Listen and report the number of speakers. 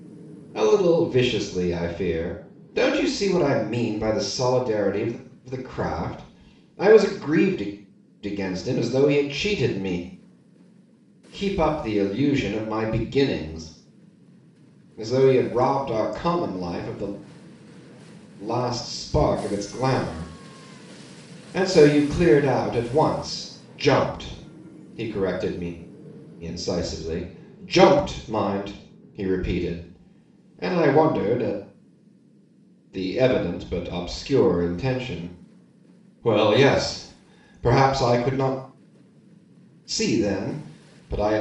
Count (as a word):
one